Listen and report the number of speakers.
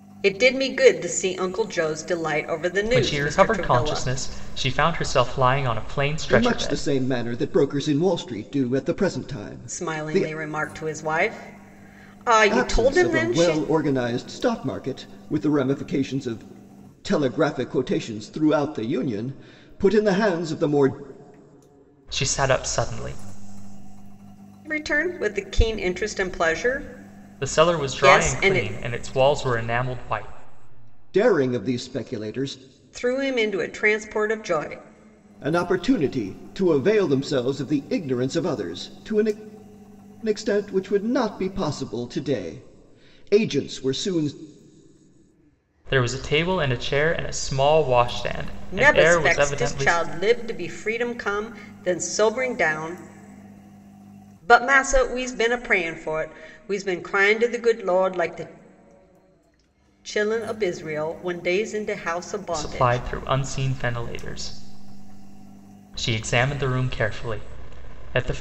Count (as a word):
three